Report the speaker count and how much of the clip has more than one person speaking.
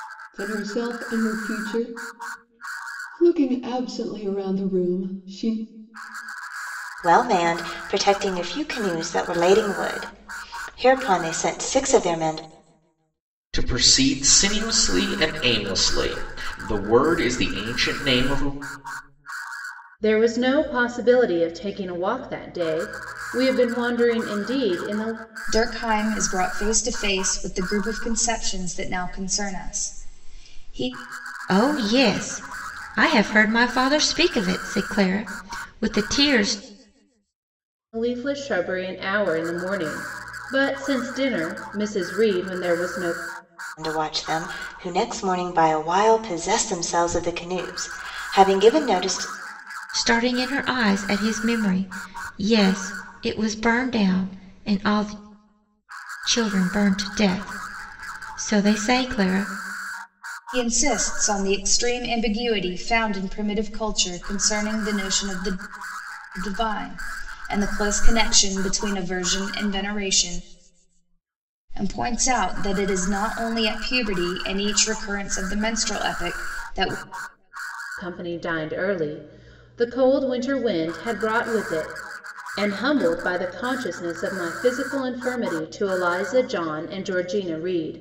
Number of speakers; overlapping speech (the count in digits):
6, no overlap